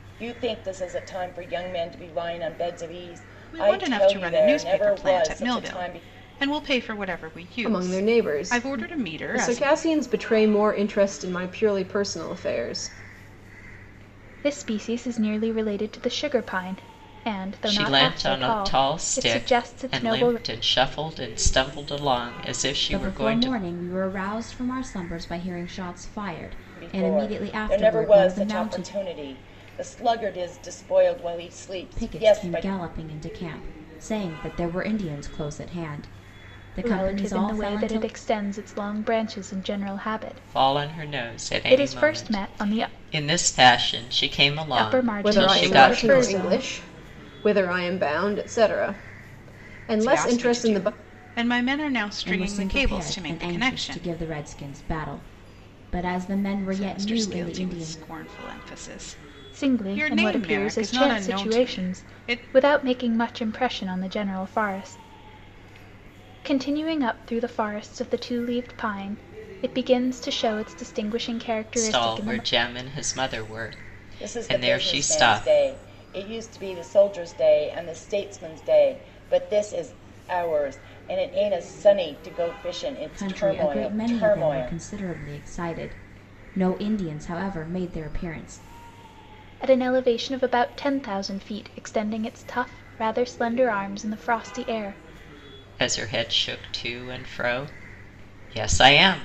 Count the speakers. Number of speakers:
6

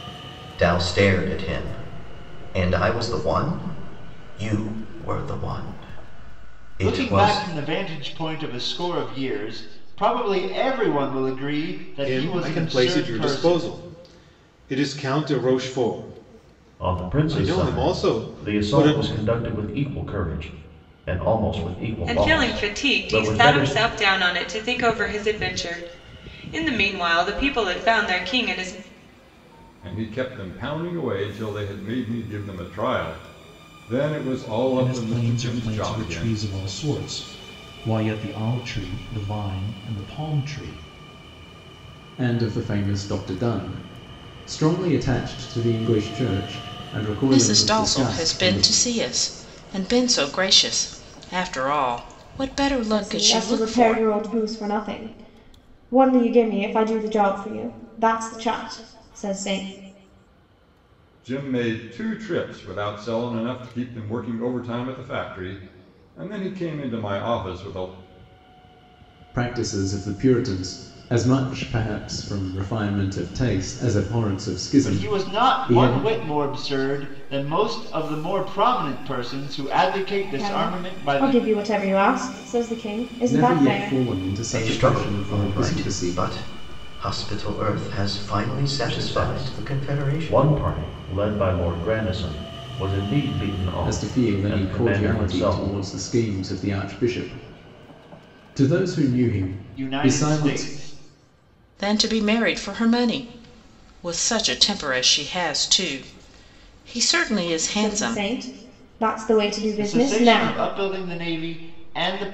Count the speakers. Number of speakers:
10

